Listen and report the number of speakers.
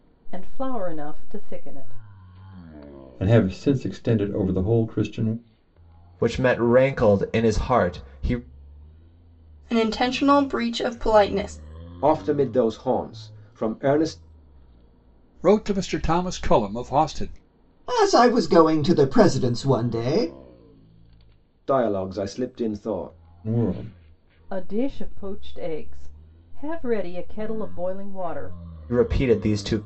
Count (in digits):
7